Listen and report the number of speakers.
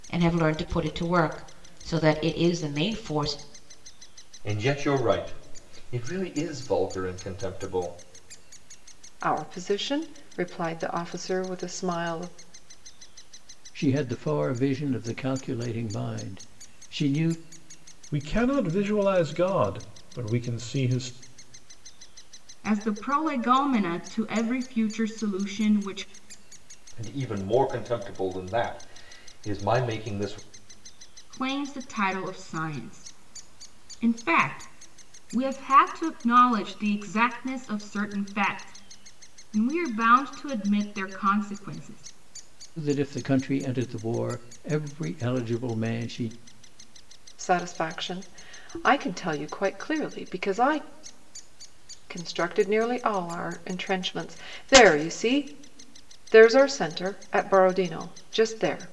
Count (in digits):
6